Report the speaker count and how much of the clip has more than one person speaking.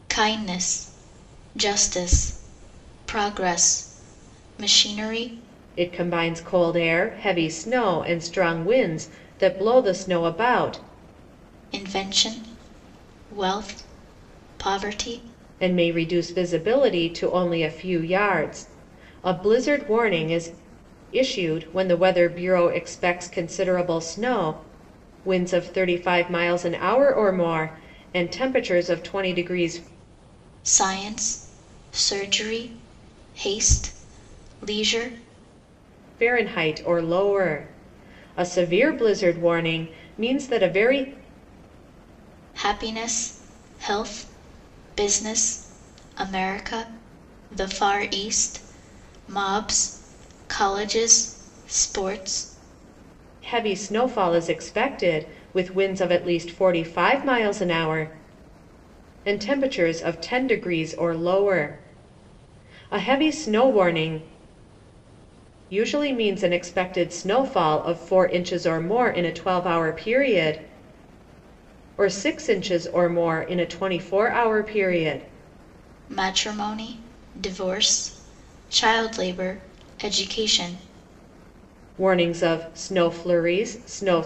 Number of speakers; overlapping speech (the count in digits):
2, no overlap